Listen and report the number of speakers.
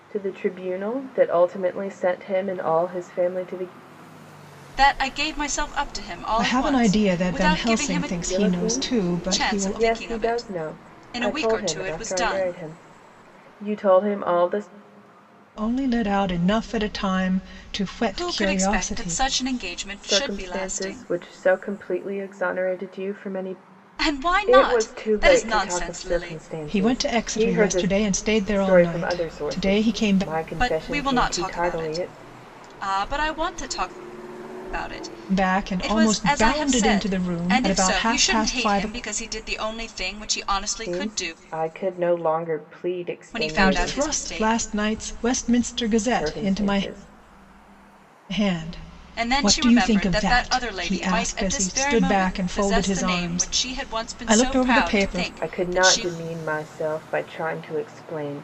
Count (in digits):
3